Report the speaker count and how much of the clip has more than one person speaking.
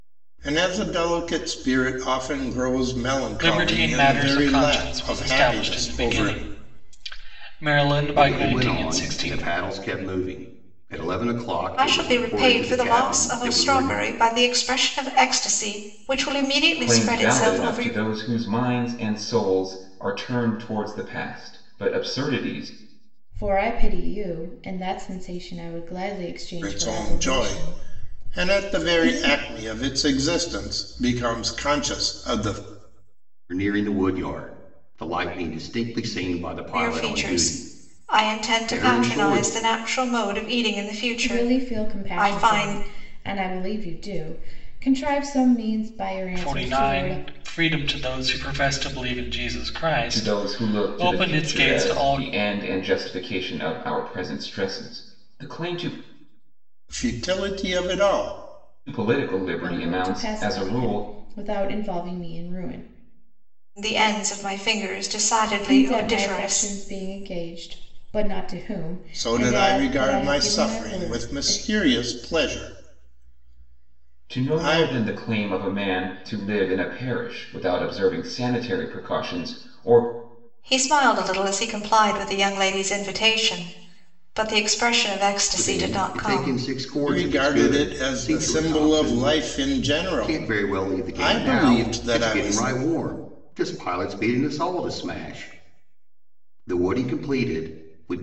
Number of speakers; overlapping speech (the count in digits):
6, about 30%